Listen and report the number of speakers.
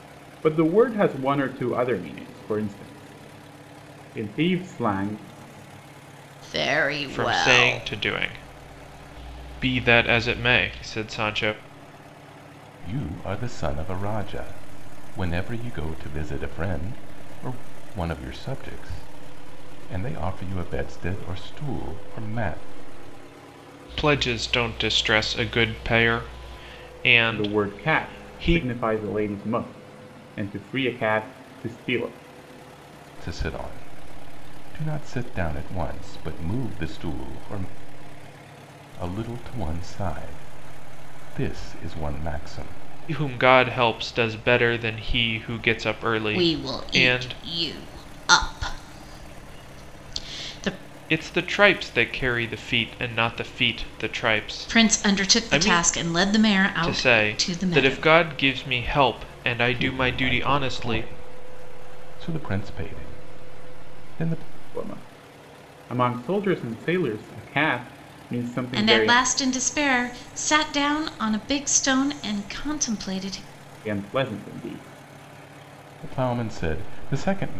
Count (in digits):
4